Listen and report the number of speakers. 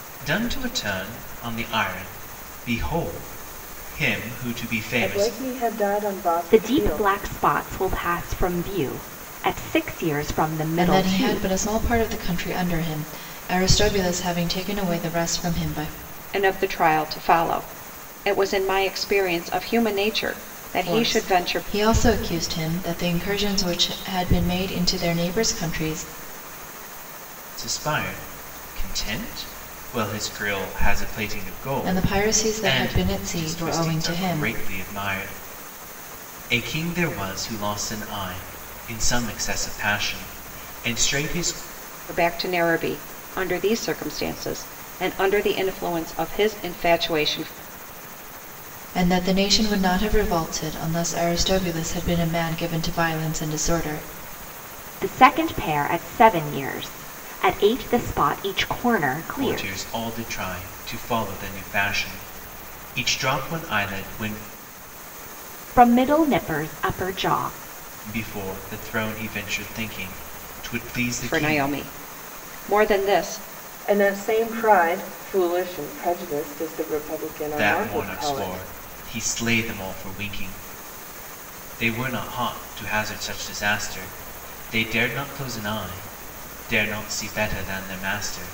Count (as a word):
five